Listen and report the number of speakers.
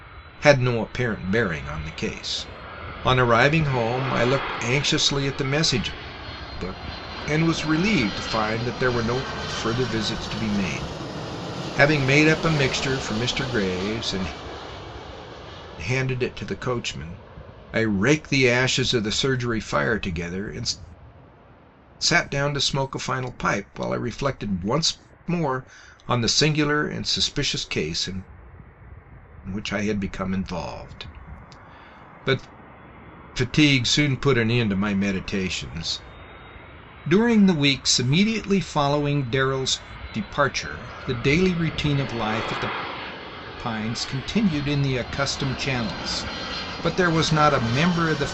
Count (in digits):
1